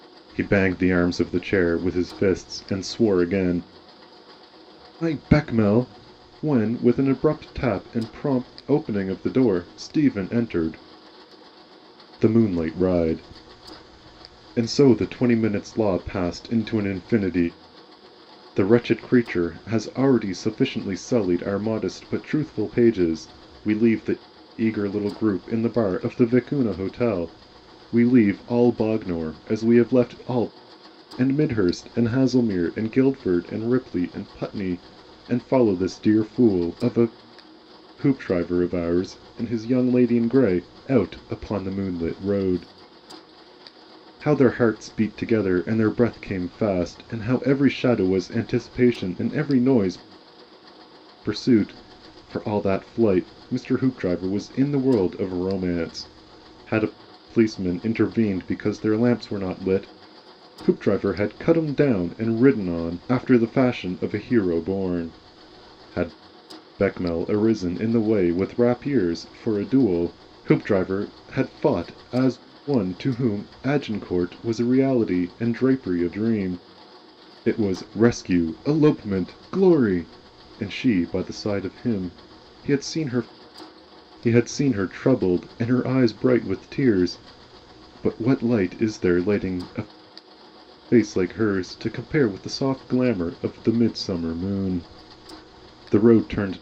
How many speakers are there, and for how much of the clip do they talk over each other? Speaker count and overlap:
1, no overlap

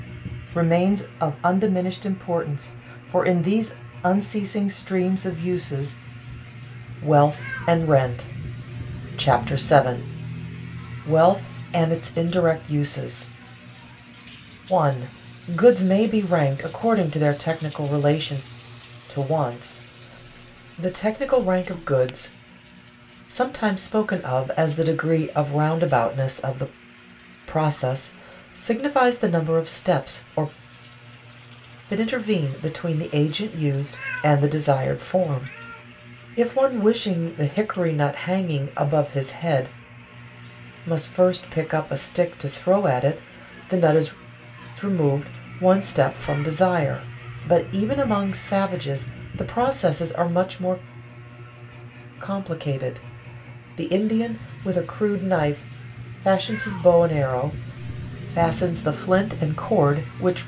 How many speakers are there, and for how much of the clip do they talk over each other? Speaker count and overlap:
1, no overlap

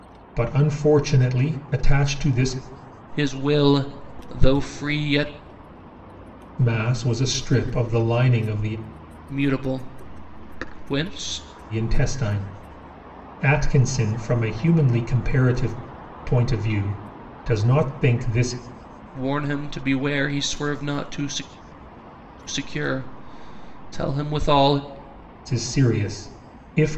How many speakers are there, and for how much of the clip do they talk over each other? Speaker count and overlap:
2, no overlap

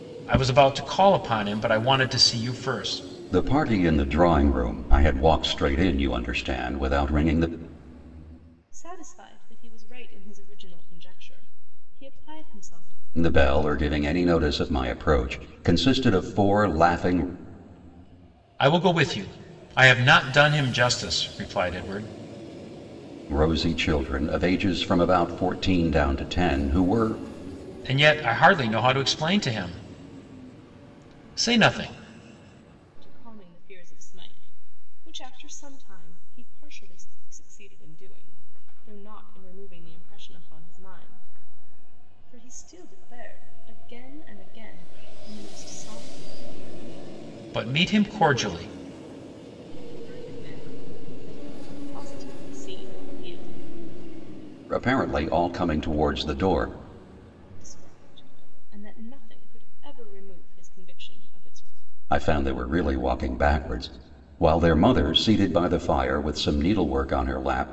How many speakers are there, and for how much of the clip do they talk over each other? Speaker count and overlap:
3, no overlap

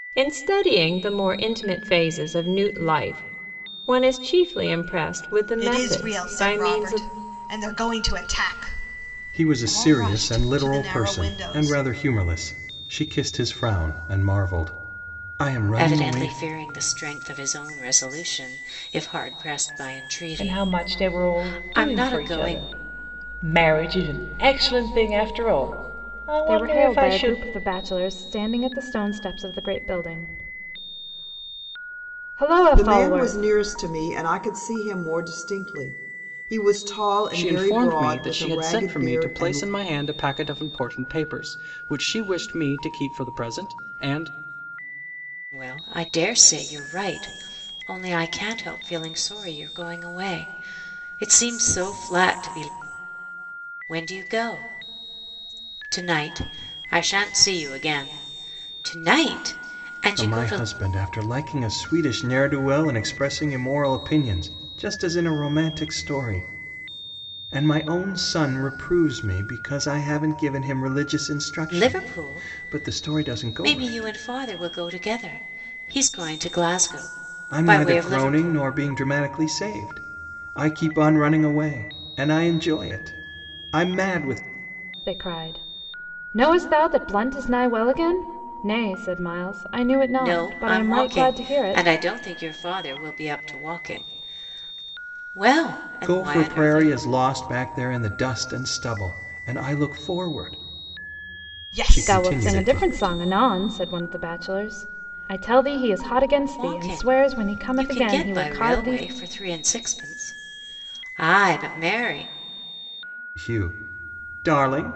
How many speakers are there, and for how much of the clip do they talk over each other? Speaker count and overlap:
8, about 19%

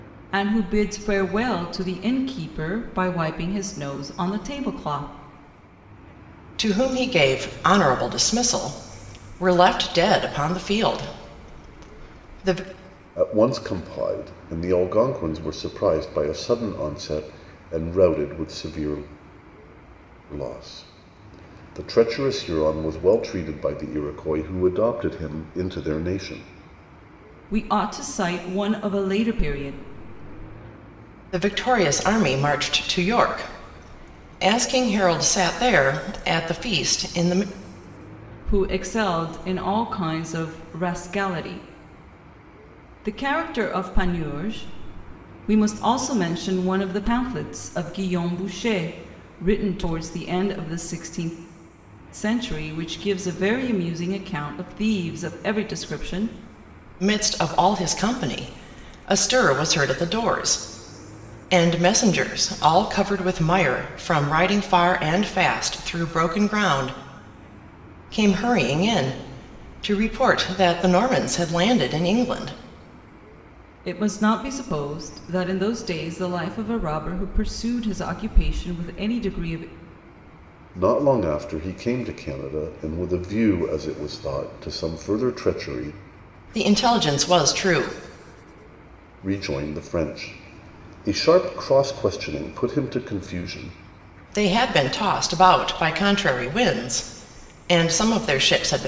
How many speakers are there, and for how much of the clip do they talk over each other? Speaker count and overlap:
3, no overlap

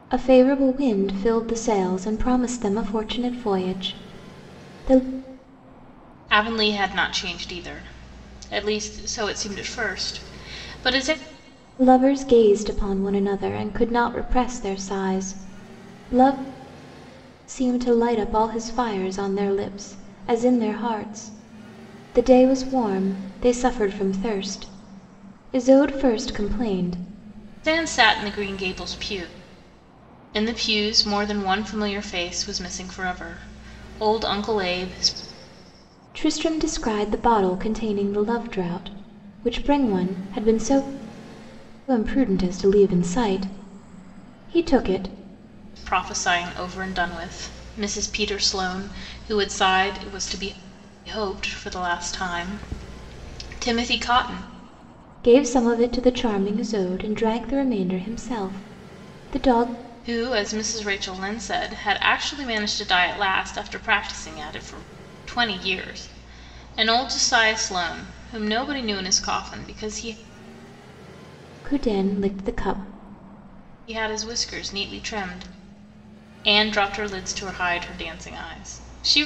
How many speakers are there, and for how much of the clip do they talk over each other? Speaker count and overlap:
2, no overlap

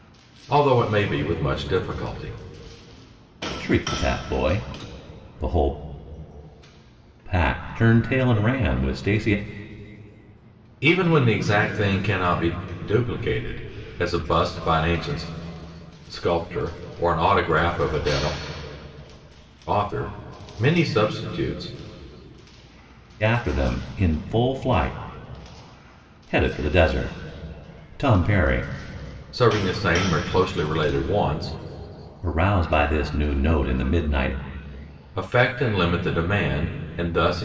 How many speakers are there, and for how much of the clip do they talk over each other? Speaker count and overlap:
2, no overlap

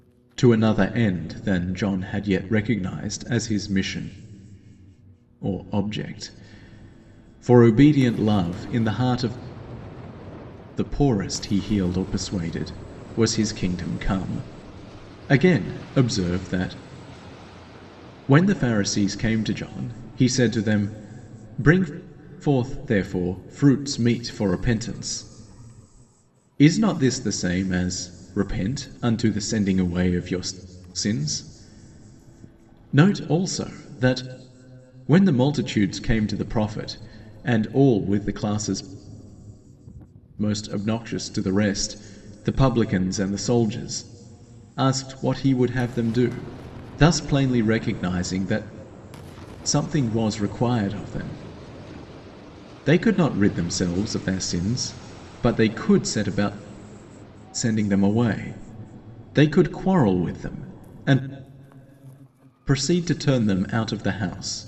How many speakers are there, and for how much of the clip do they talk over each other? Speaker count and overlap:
1, no overlap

